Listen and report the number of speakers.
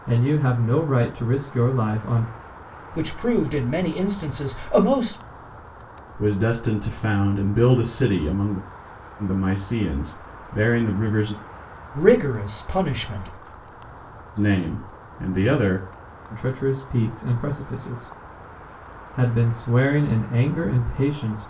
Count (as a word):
three